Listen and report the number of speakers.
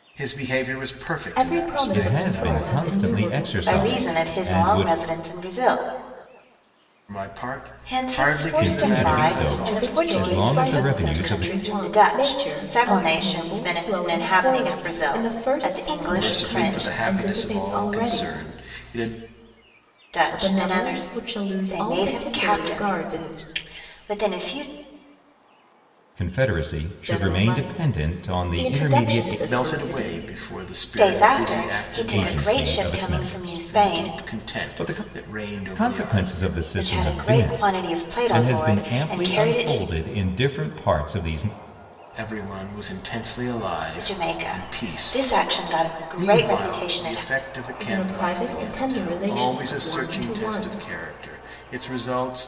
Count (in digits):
4